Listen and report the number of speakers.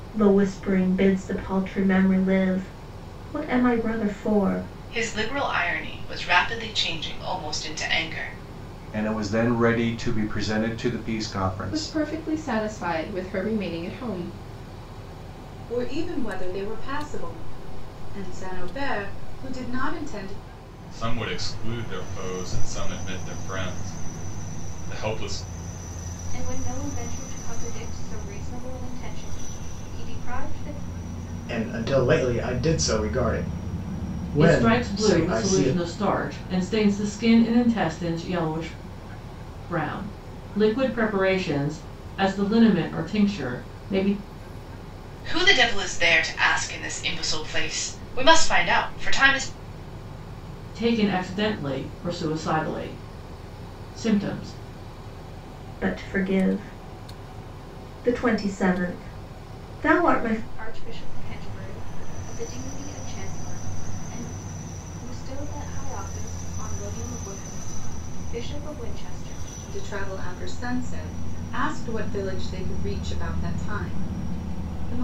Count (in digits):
9